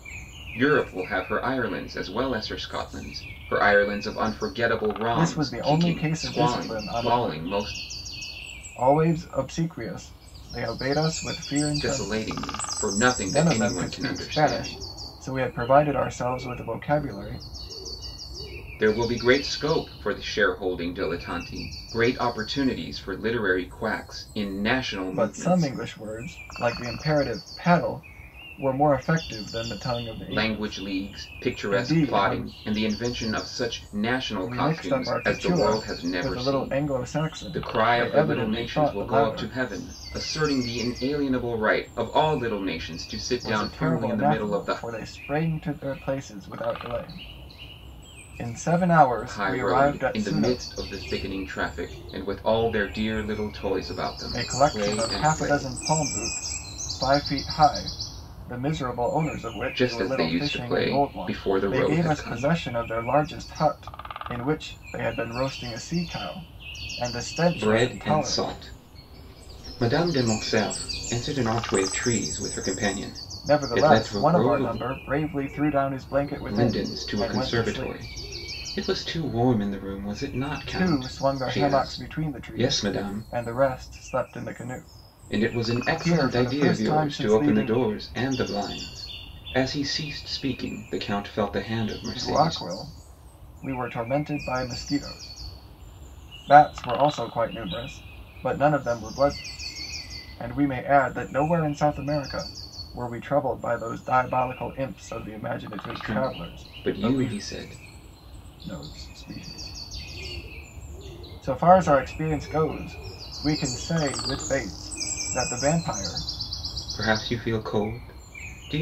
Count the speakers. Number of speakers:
2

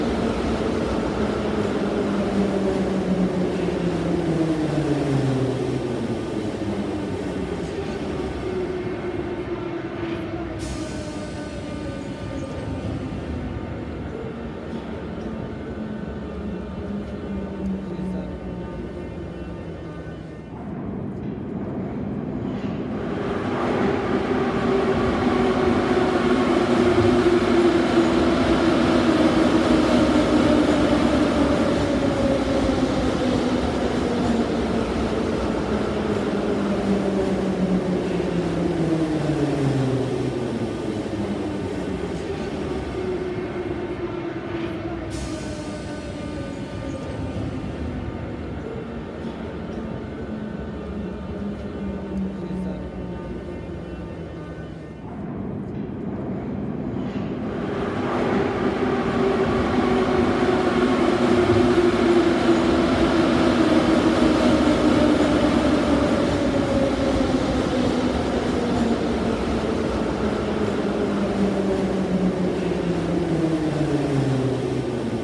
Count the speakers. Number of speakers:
0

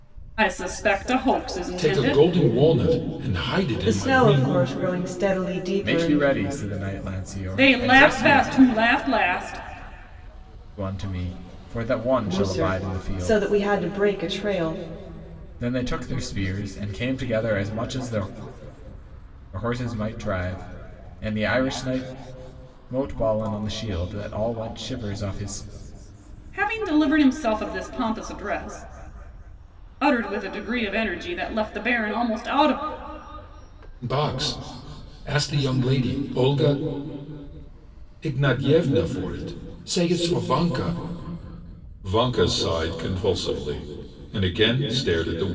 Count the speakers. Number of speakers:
4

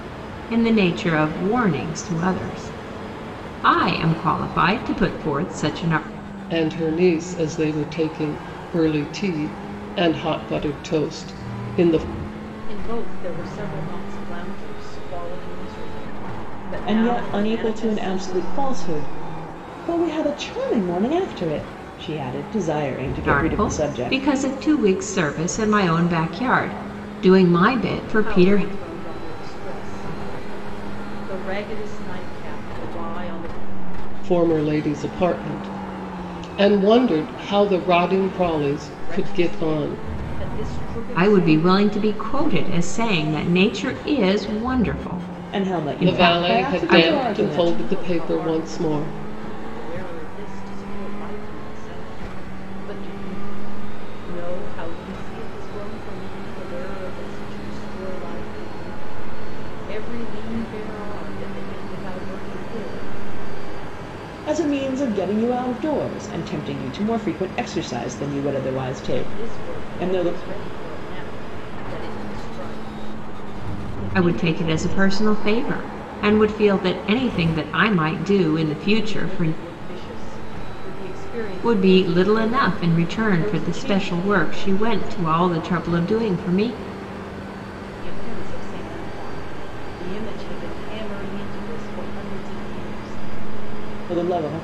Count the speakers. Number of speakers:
4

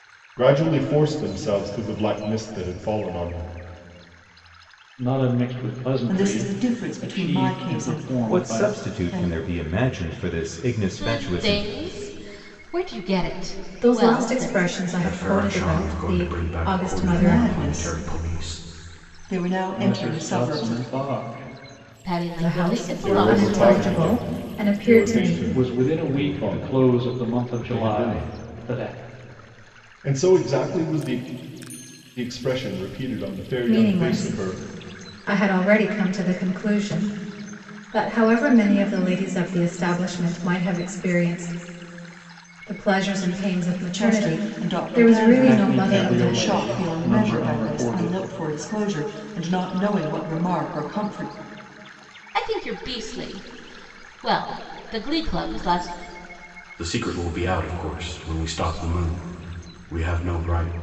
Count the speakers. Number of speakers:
7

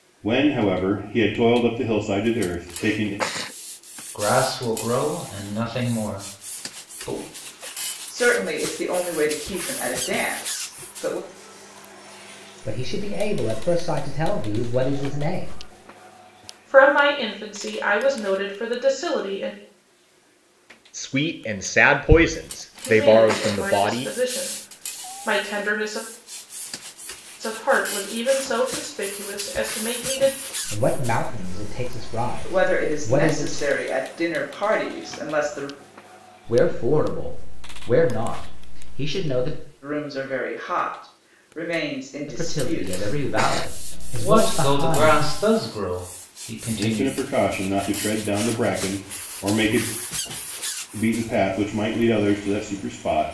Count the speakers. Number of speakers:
6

